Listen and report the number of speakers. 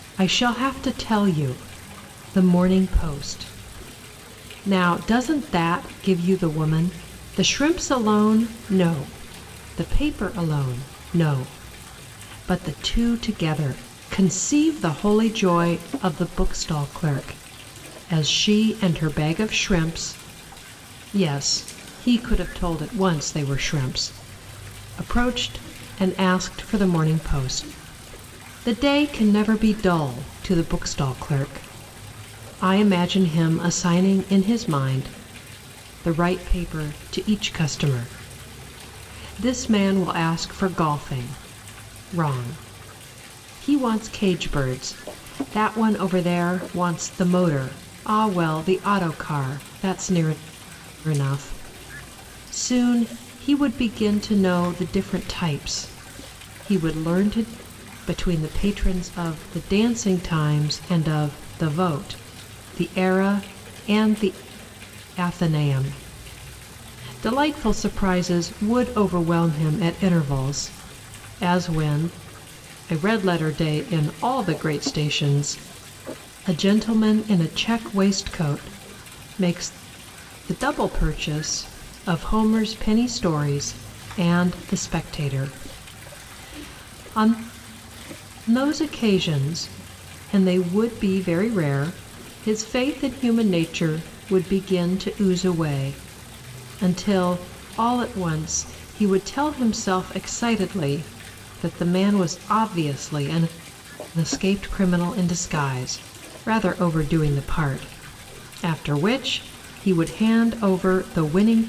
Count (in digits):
1